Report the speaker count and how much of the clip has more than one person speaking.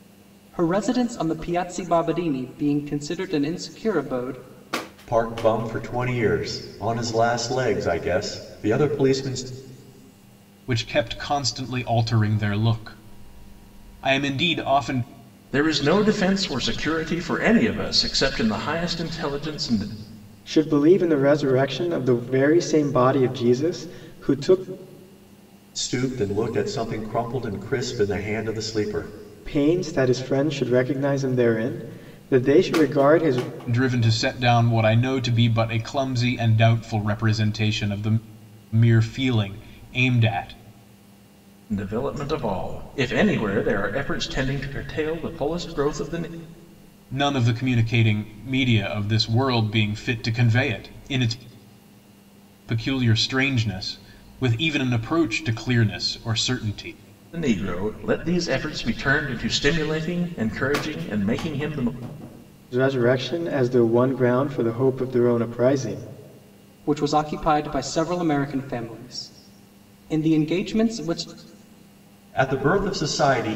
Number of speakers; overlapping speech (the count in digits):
5, no overlap